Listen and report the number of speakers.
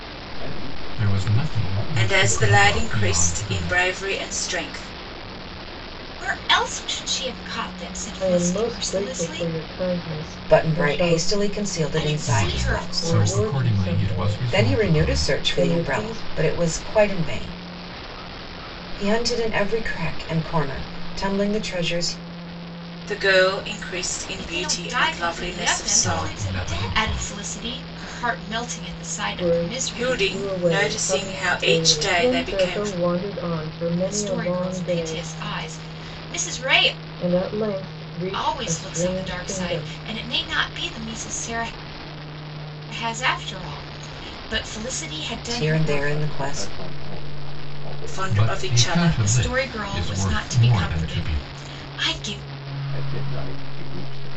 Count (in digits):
6